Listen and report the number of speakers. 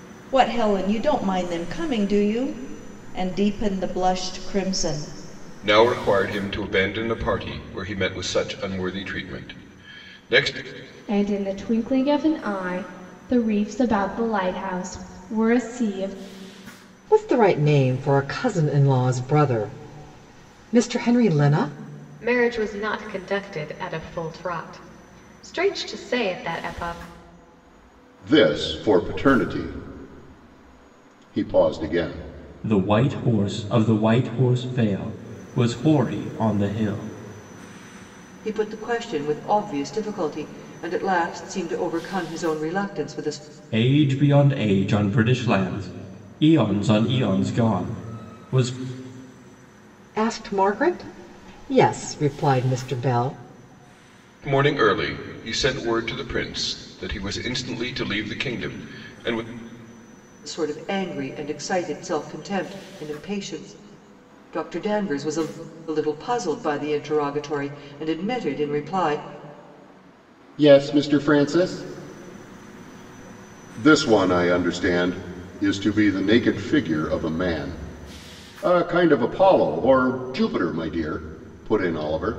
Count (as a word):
eight